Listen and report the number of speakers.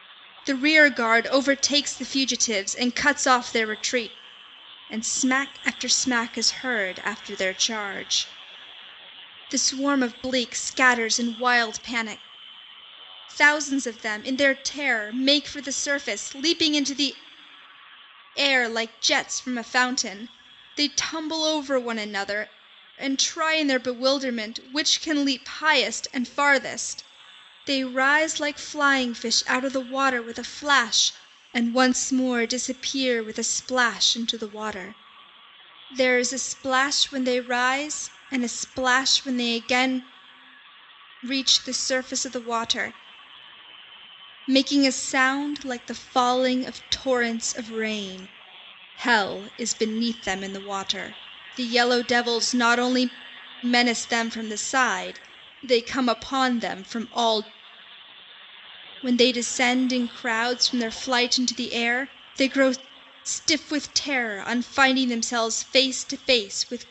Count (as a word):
one